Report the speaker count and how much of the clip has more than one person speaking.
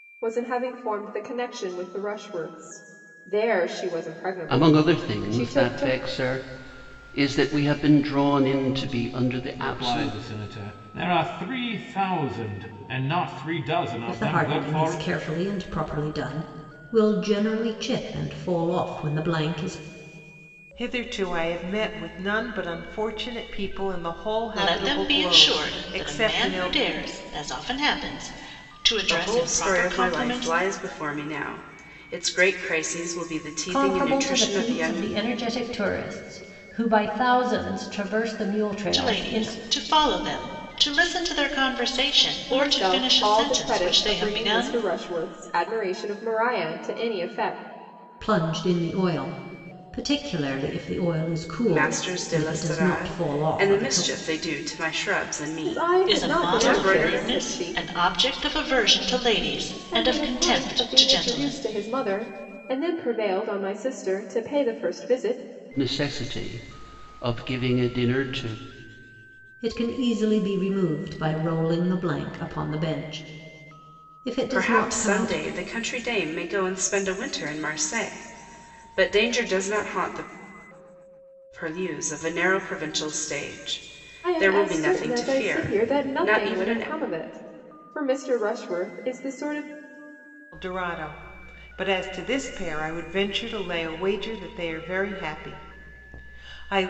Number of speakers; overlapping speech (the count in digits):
8, about 22%